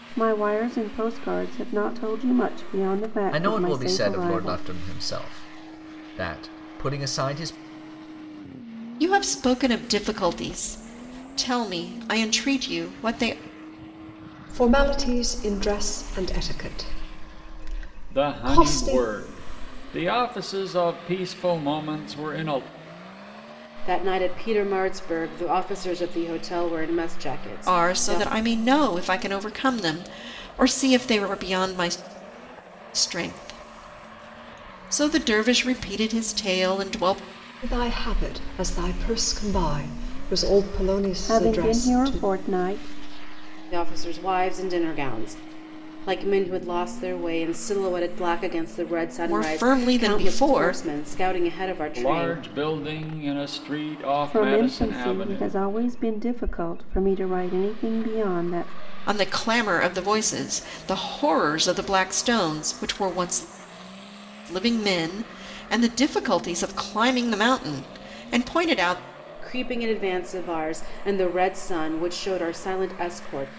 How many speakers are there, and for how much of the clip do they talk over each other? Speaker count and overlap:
six, about 10%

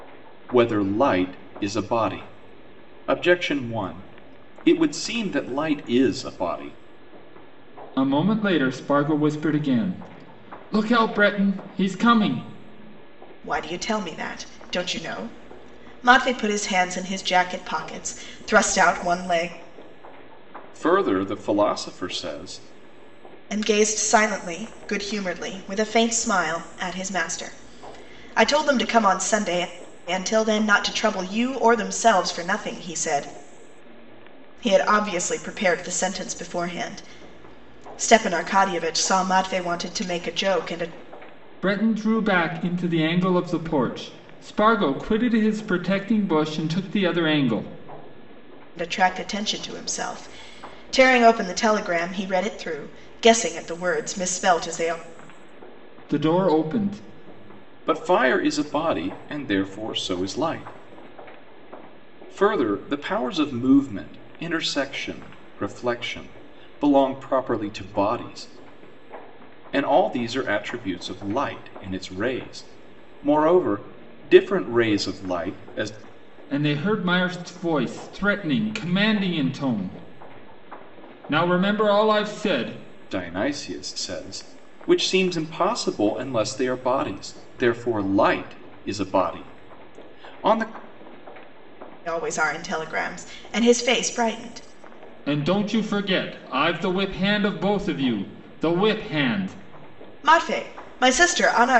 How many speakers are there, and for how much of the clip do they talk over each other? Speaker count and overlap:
three, no overlap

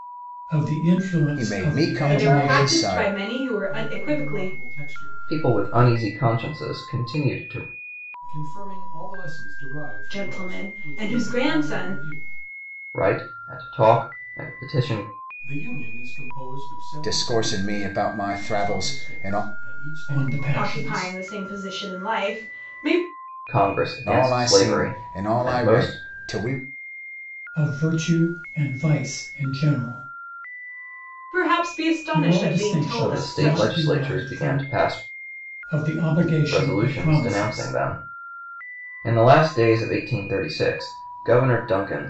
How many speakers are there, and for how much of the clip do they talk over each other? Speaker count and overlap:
five, about 34%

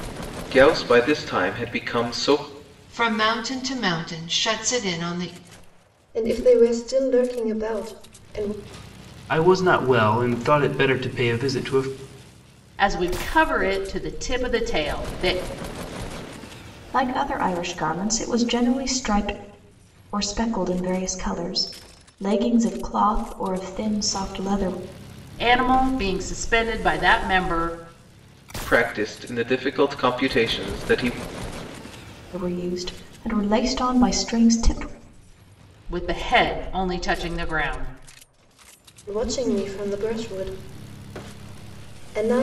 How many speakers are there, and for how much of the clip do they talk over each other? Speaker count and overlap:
six, no overlap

